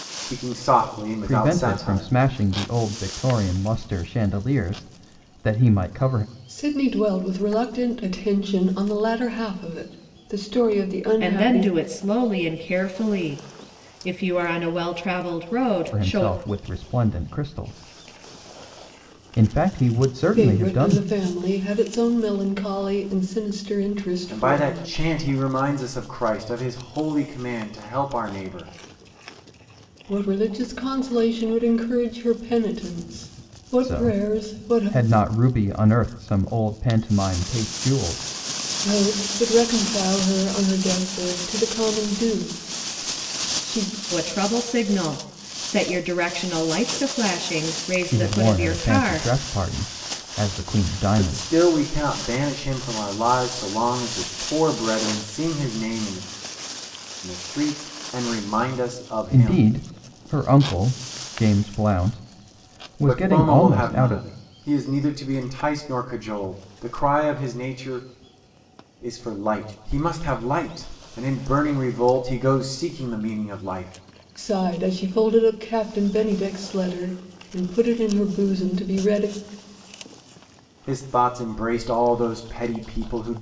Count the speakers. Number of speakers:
4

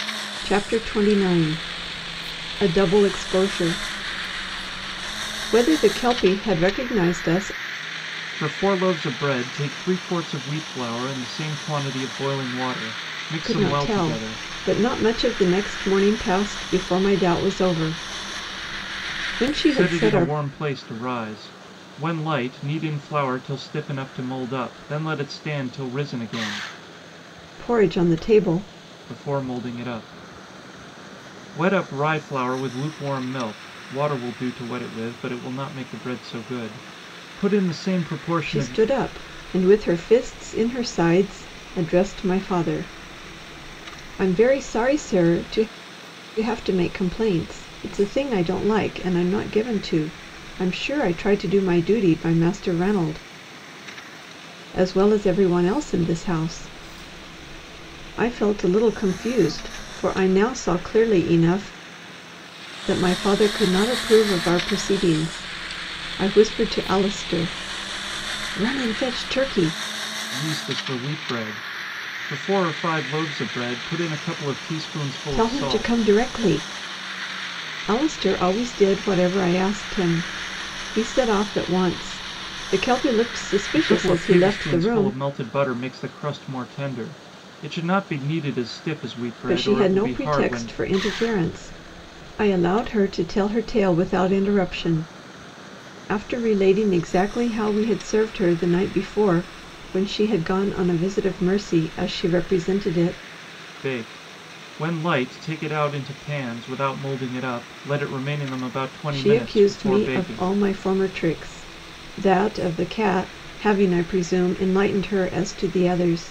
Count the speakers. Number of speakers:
2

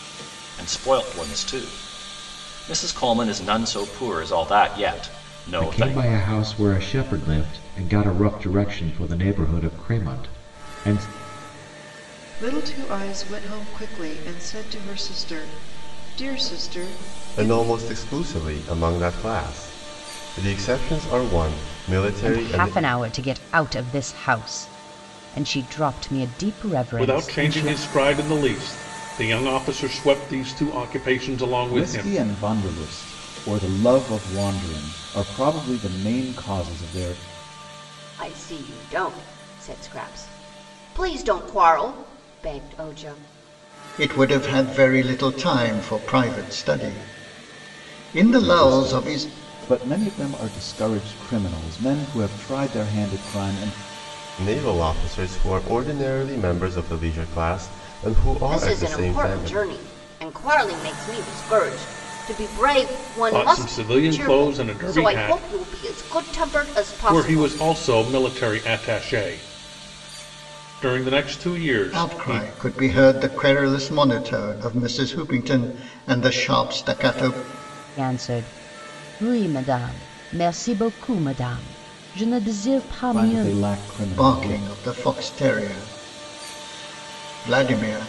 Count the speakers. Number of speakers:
9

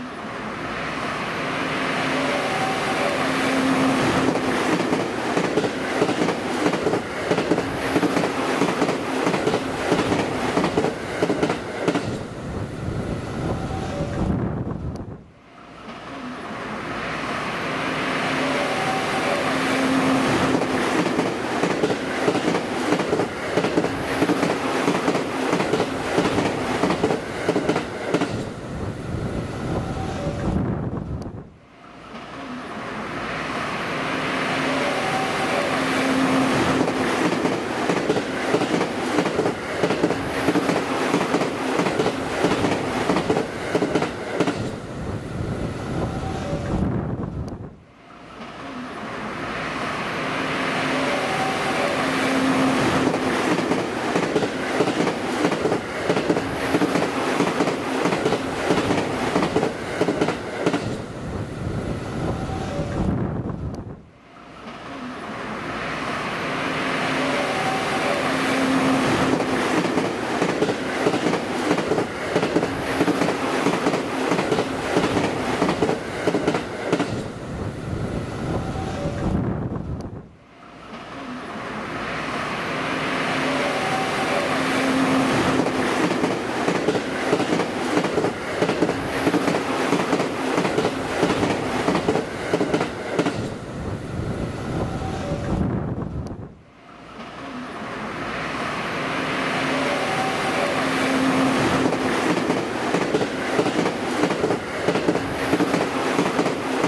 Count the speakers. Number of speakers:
0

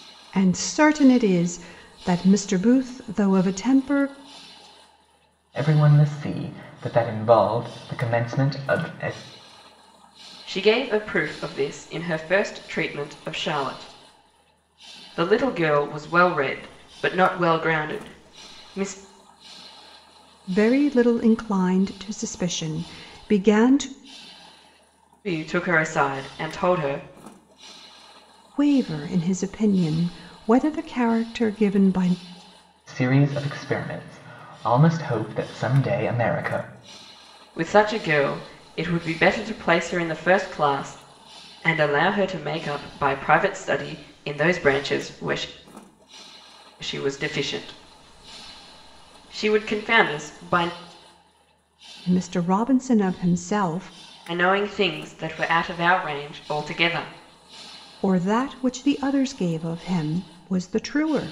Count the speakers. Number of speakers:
3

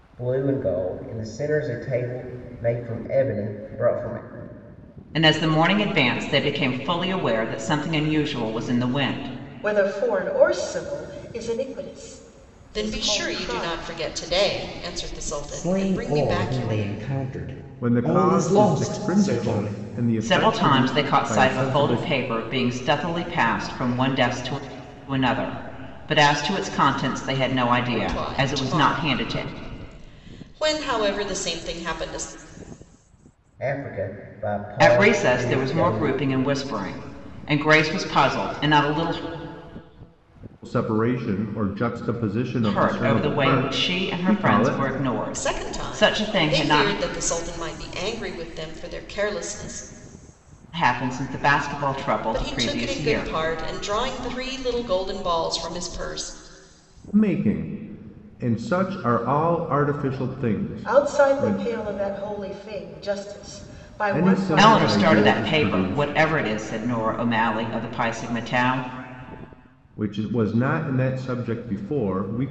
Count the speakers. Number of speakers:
6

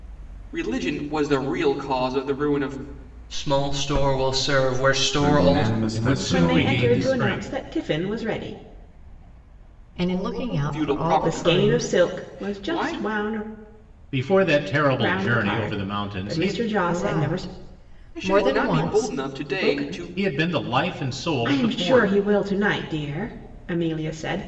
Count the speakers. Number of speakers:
6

